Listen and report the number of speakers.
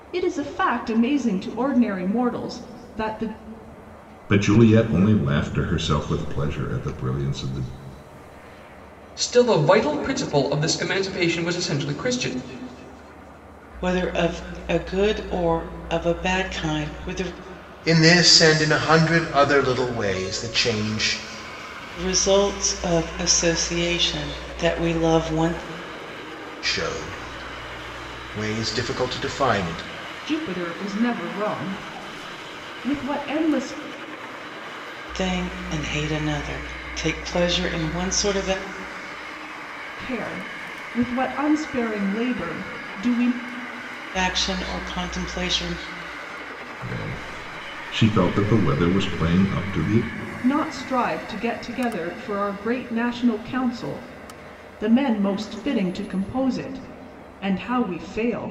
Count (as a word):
five